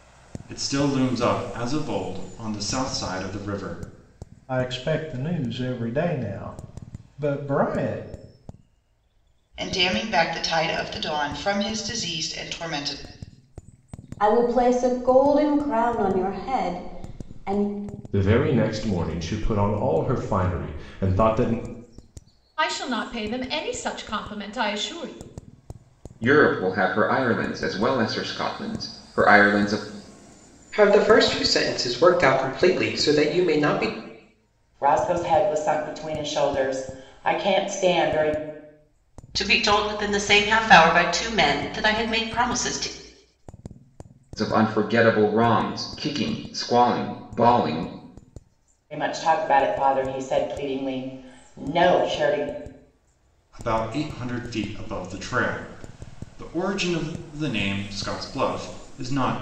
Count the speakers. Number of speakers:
ten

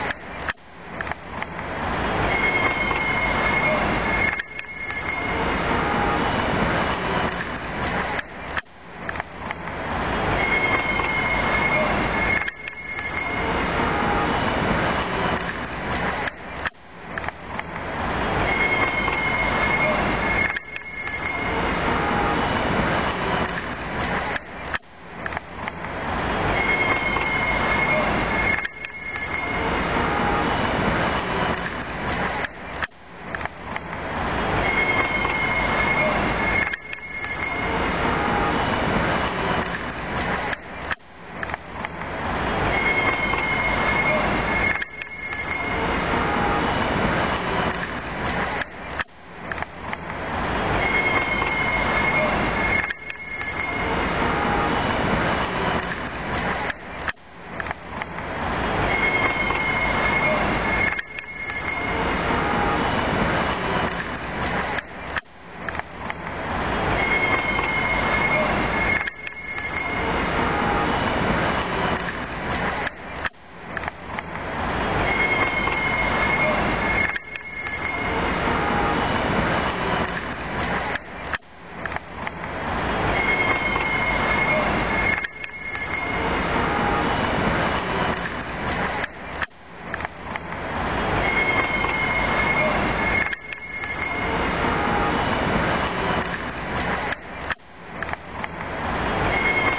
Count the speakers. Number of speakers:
zero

